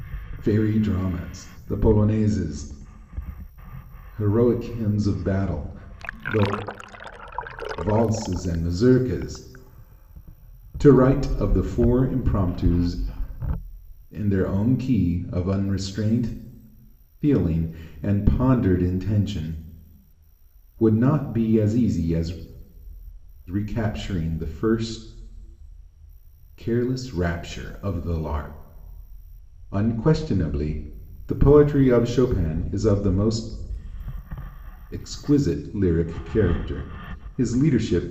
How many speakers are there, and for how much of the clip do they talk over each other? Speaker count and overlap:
one, no overlap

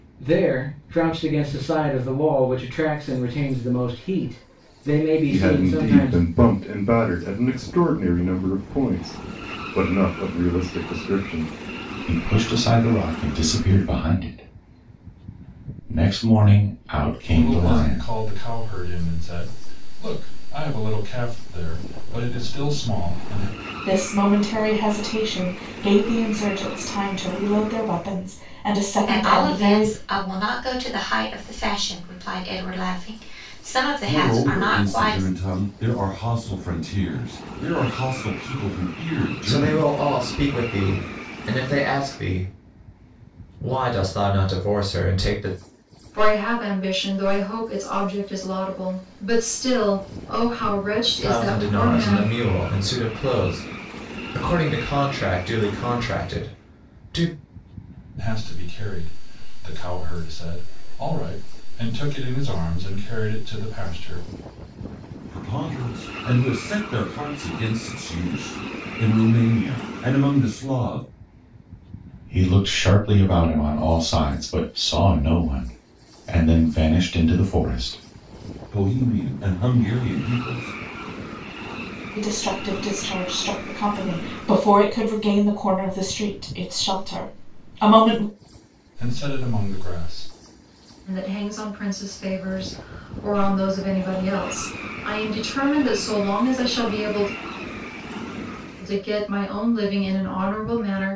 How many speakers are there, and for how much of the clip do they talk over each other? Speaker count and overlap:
nine, about 6%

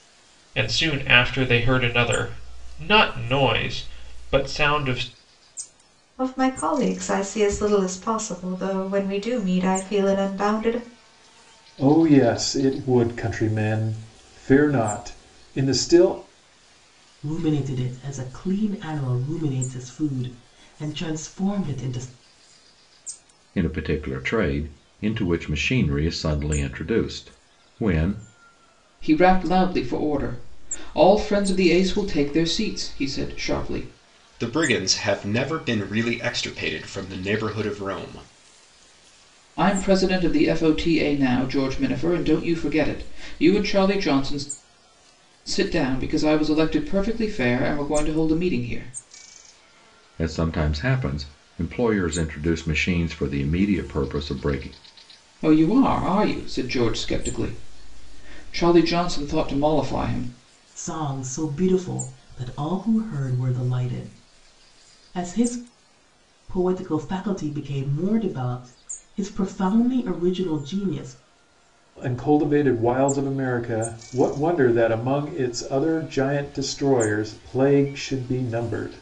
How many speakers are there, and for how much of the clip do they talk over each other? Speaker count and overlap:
seven, no overlap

